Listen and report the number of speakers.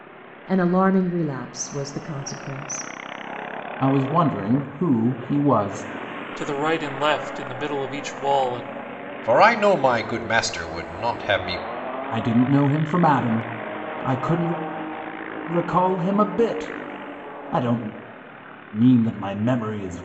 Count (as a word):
four